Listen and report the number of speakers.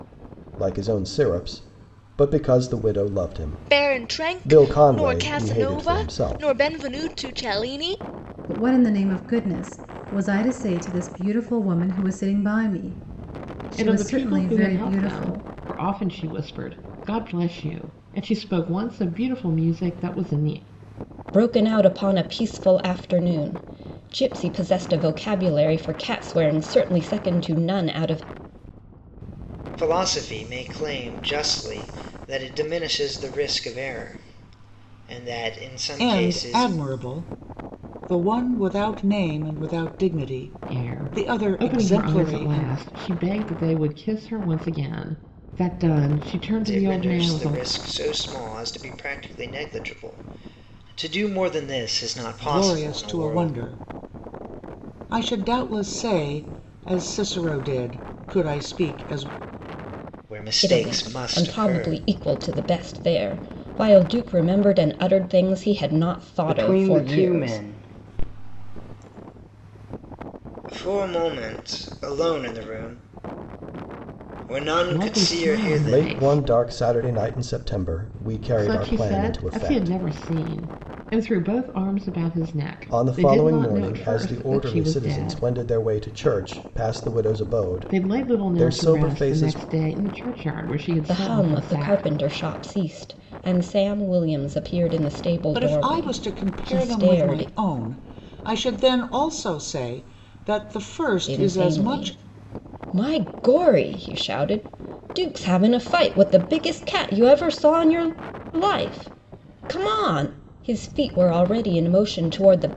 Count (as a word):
seven